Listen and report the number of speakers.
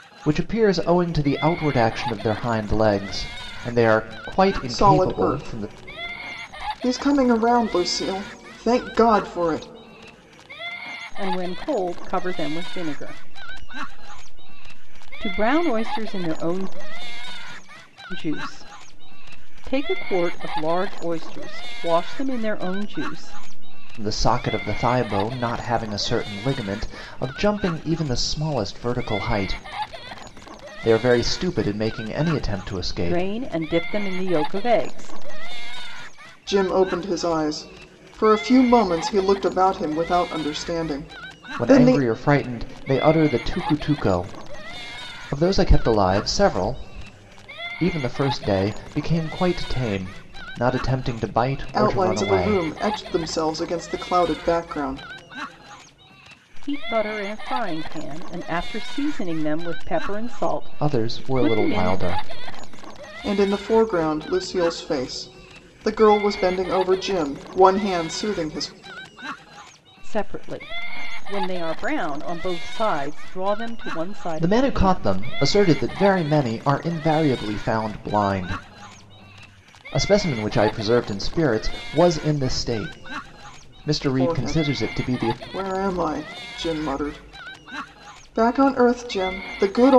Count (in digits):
3